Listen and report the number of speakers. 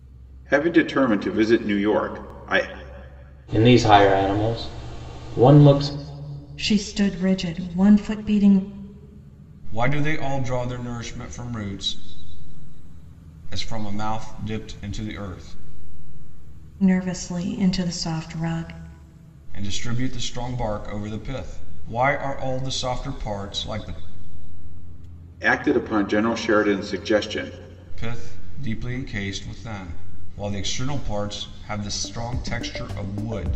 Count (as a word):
four